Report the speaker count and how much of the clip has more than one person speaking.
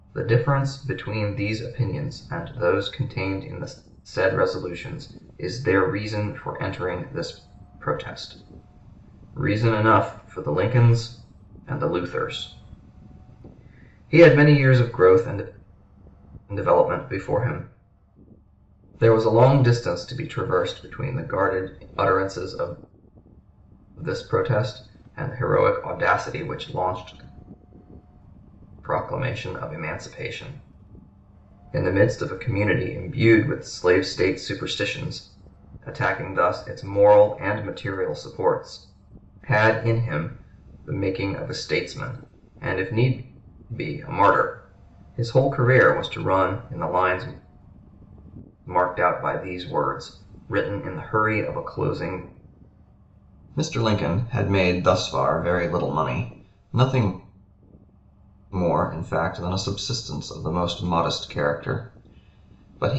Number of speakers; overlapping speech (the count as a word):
one, no overlap